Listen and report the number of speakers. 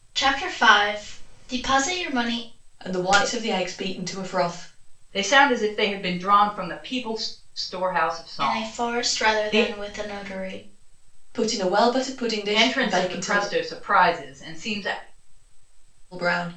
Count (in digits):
3